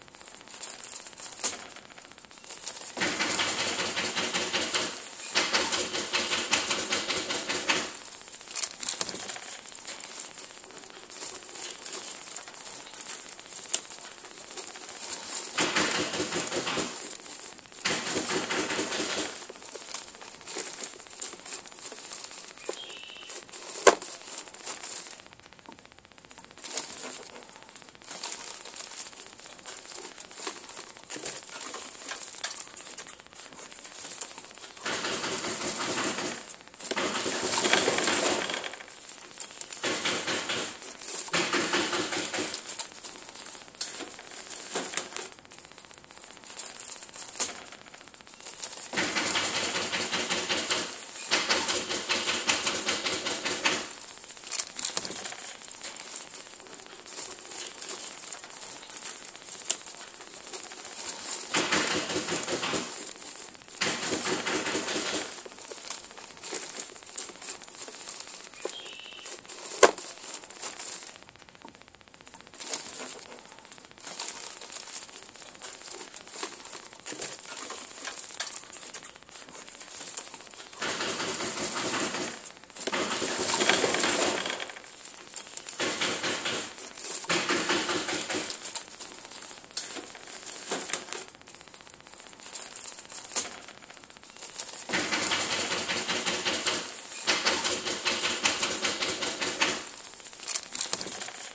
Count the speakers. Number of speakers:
zero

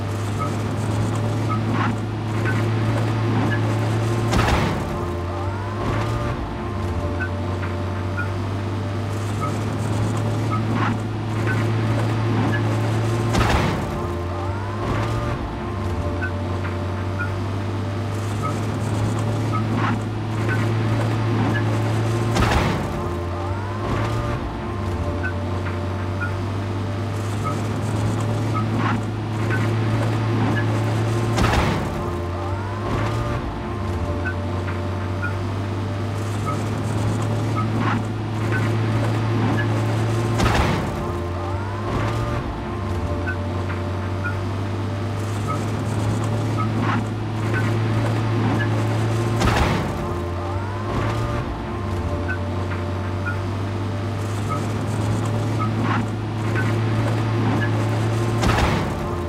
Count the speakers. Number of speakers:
zero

